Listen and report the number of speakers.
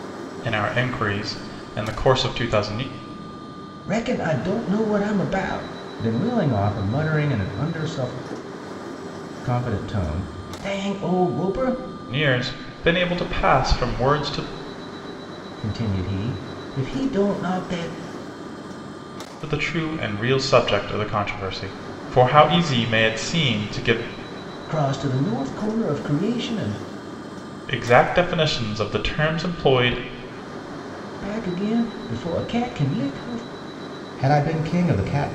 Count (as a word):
two